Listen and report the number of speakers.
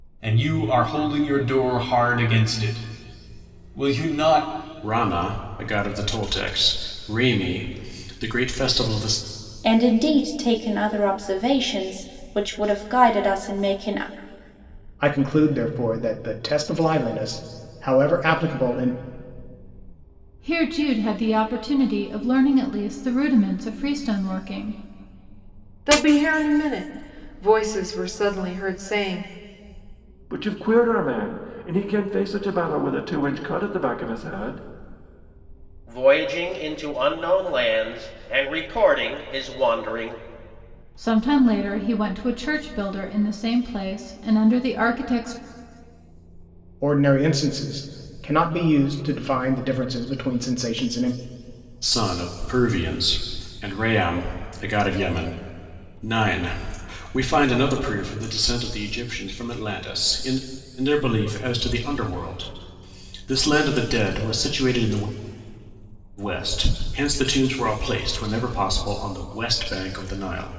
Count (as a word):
eight